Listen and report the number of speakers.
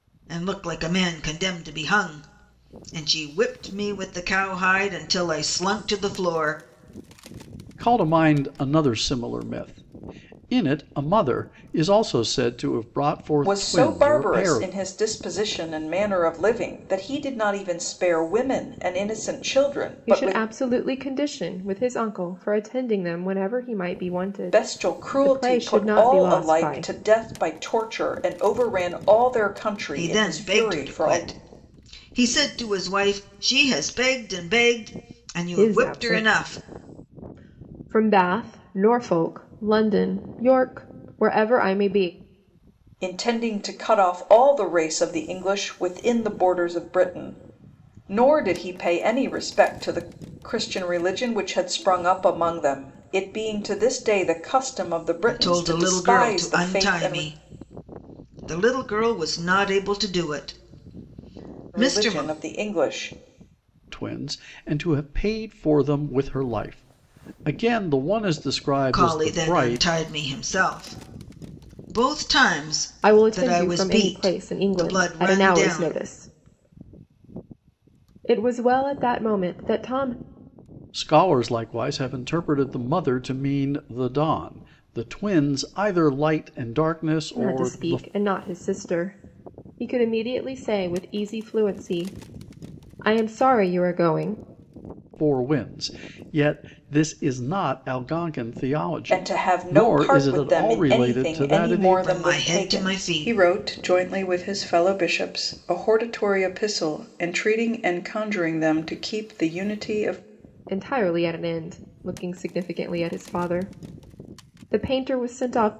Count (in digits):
4